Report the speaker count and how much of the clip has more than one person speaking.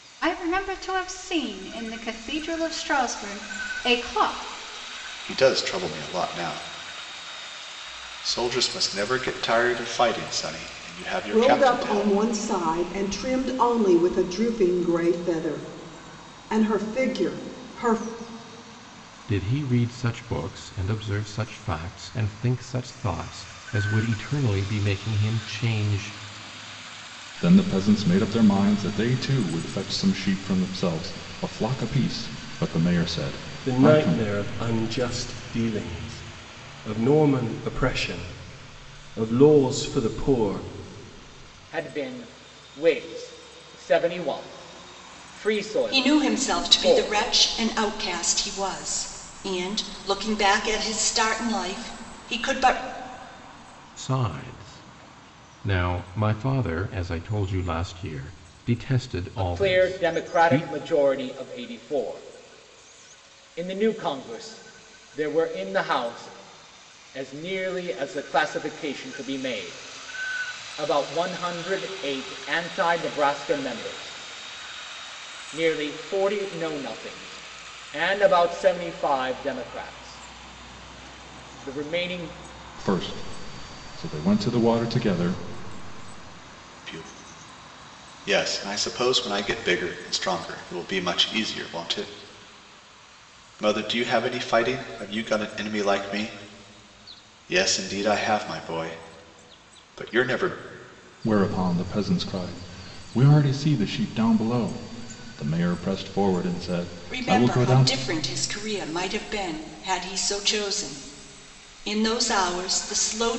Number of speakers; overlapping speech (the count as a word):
eight, about 5%